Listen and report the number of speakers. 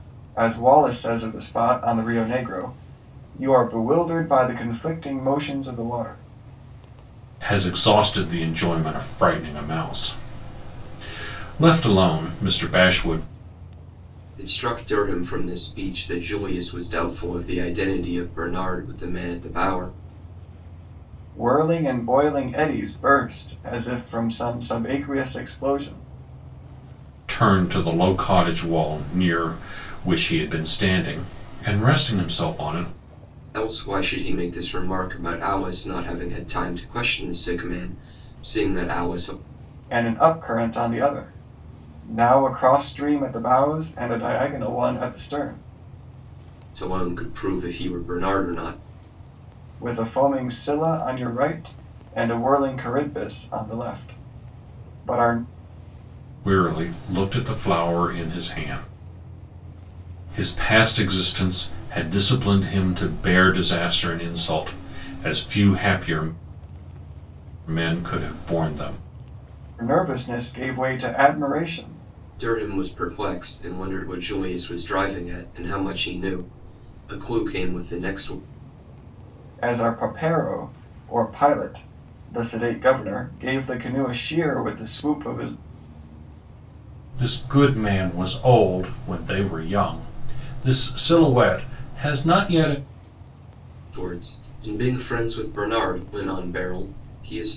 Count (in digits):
3